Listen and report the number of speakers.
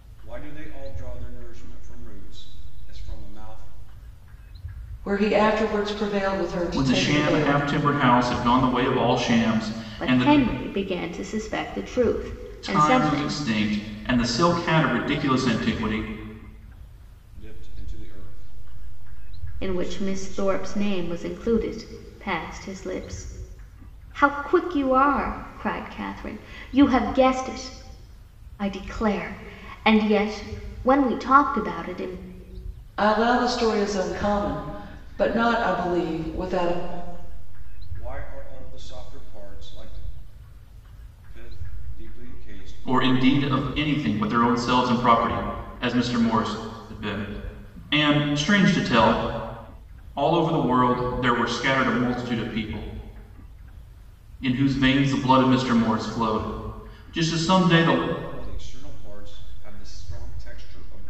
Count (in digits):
4